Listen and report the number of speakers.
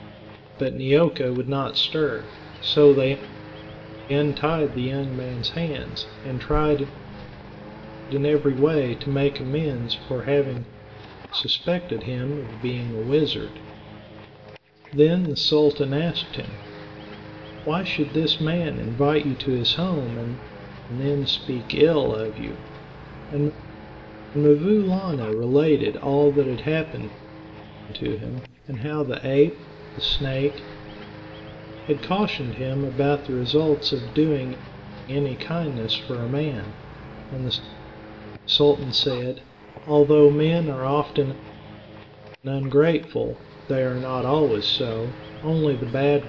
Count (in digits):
1